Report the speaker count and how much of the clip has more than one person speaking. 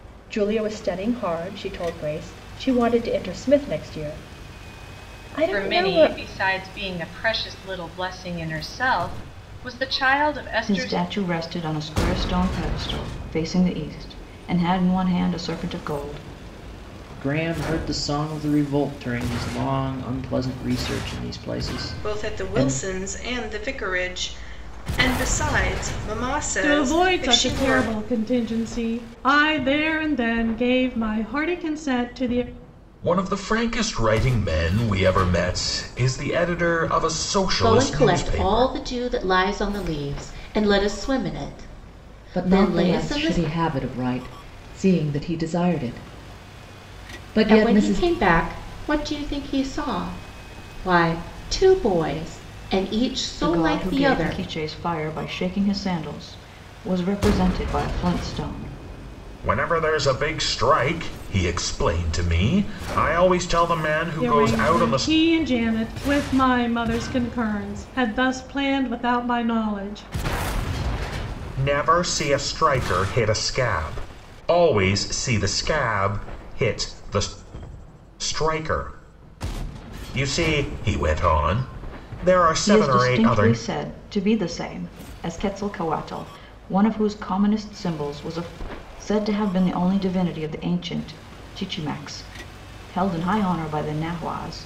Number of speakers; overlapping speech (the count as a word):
nine, about 10%